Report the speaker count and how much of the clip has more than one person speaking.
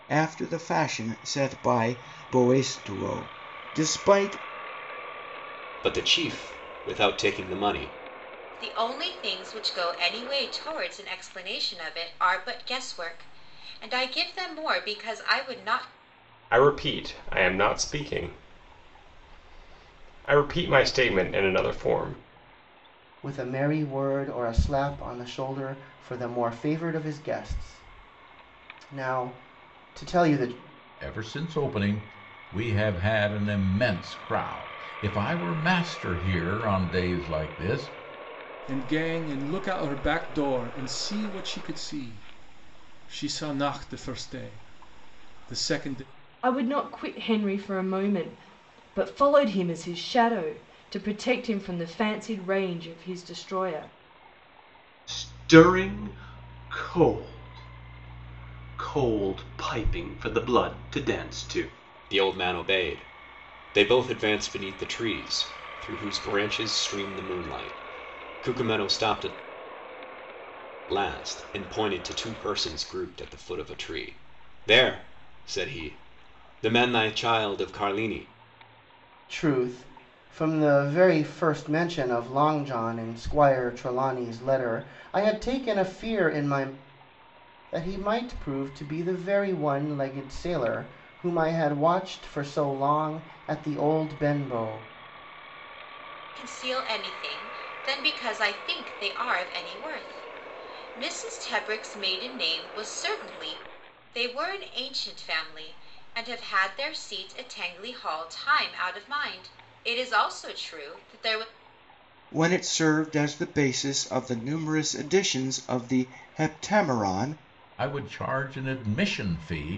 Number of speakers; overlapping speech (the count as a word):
nine, no overlap